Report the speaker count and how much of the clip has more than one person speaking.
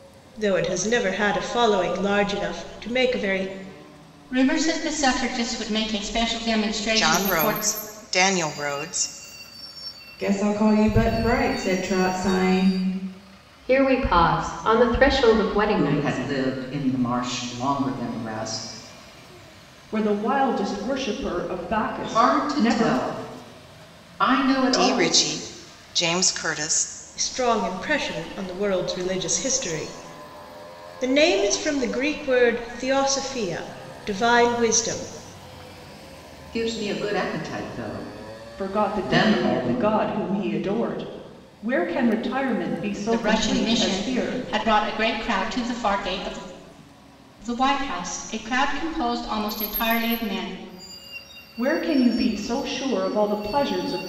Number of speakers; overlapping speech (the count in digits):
7, about 10%